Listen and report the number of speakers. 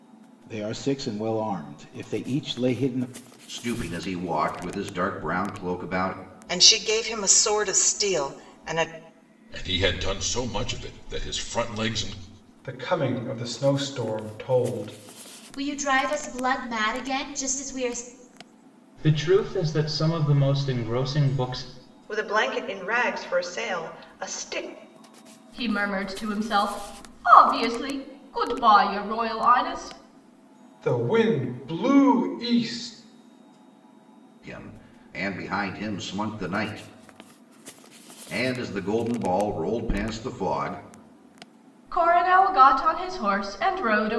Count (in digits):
9